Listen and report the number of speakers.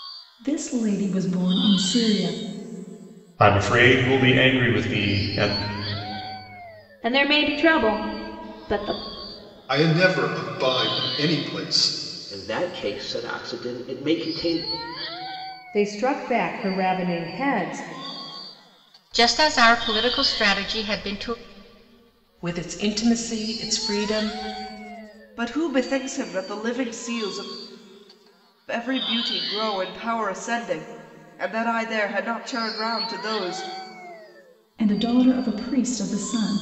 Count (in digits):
9